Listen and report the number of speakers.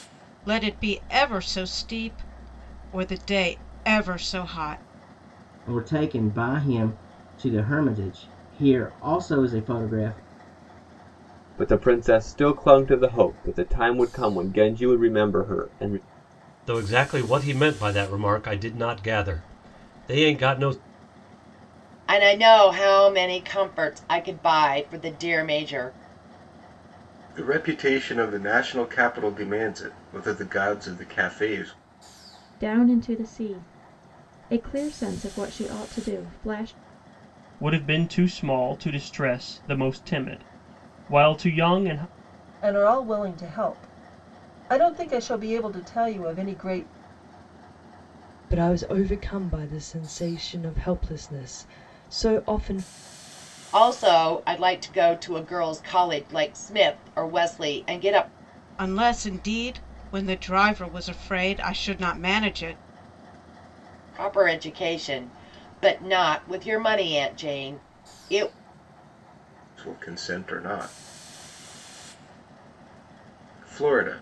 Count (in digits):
10